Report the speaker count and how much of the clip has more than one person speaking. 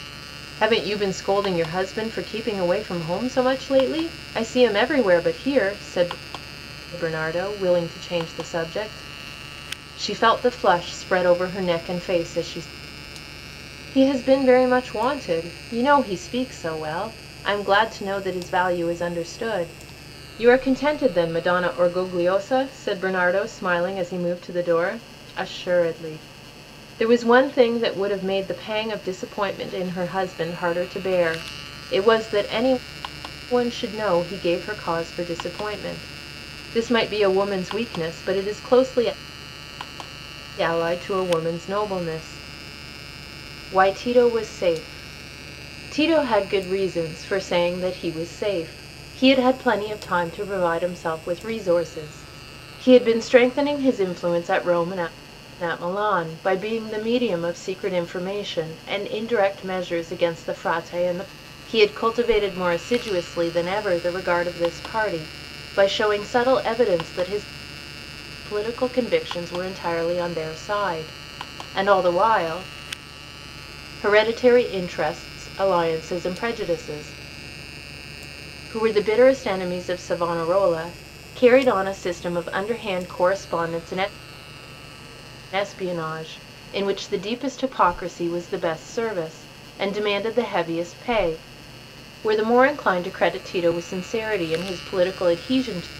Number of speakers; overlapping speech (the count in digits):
1, no overlap